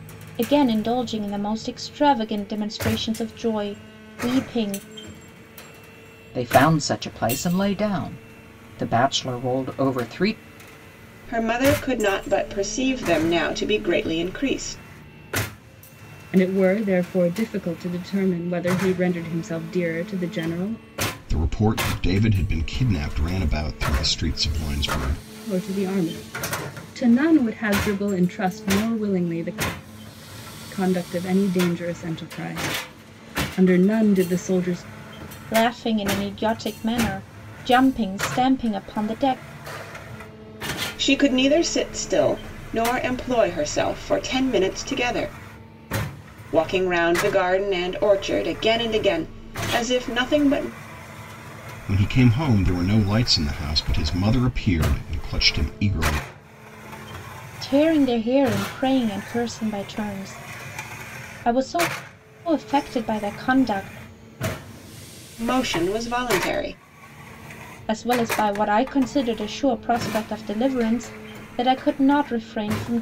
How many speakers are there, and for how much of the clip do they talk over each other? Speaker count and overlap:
5, no overlap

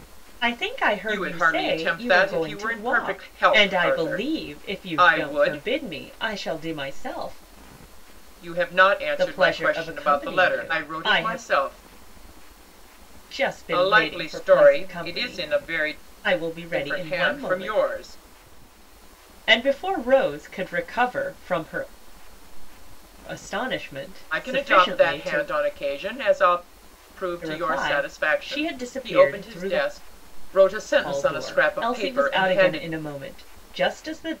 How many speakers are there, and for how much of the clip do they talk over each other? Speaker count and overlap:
2, about 45%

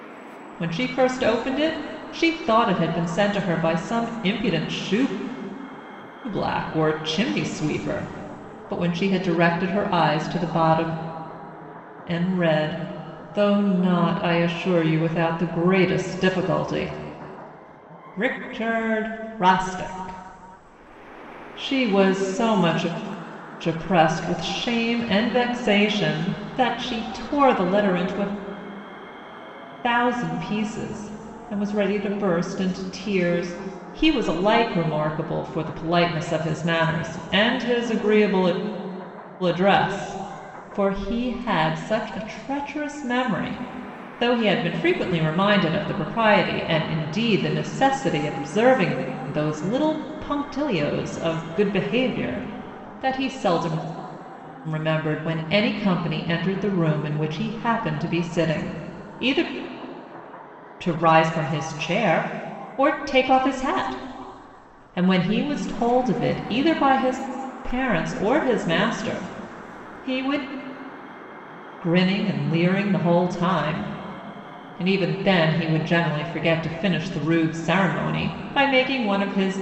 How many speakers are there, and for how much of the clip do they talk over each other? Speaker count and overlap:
1, no overlap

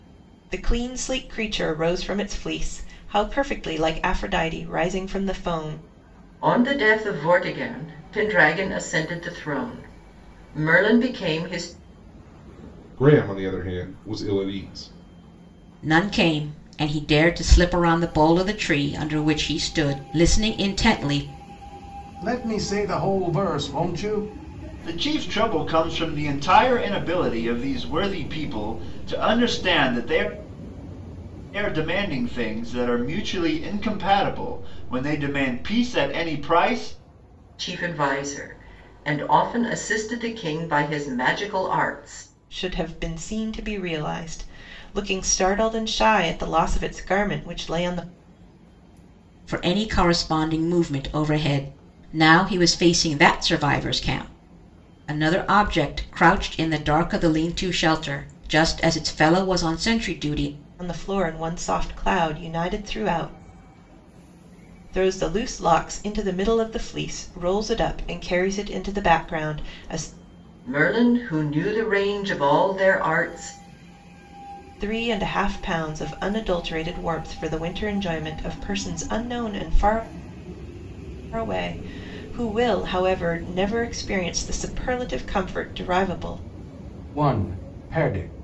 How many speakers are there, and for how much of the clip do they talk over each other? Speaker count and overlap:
6, no overlap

